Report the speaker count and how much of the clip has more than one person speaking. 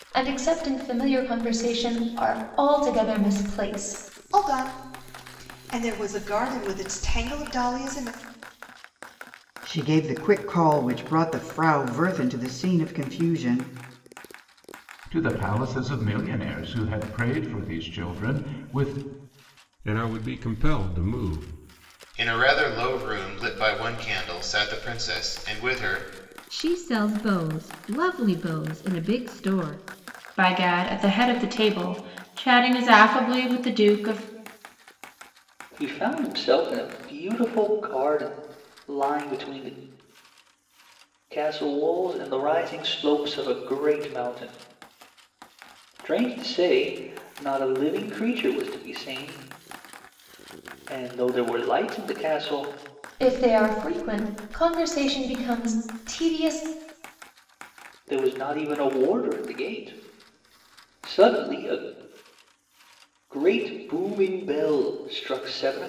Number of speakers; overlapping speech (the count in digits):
9, no overlap